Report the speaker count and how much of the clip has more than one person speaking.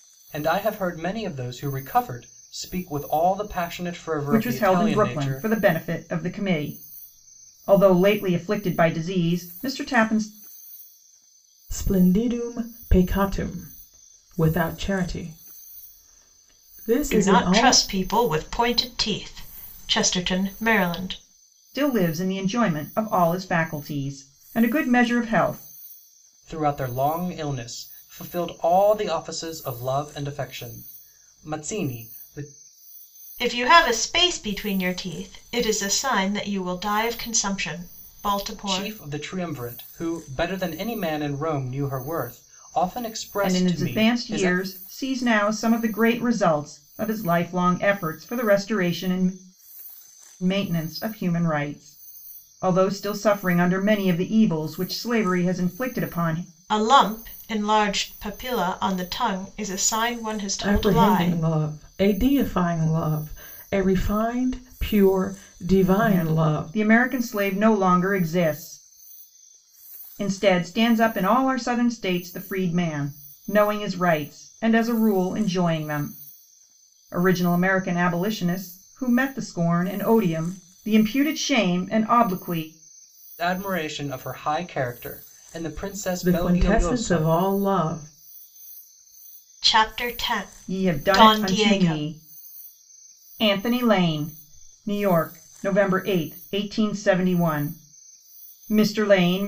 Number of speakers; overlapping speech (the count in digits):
4, about 8%